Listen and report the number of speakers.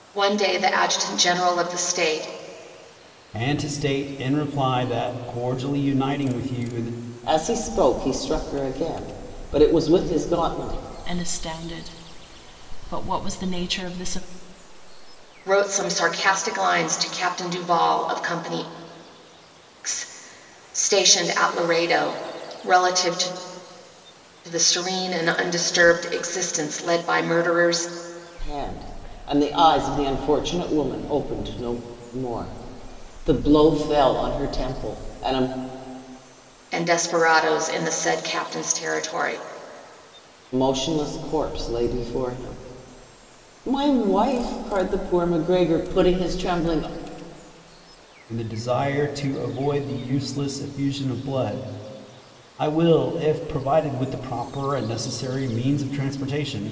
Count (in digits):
4